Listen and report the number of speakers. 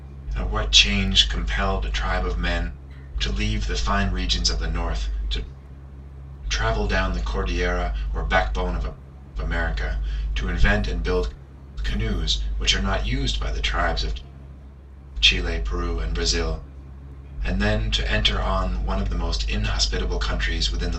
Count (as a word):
one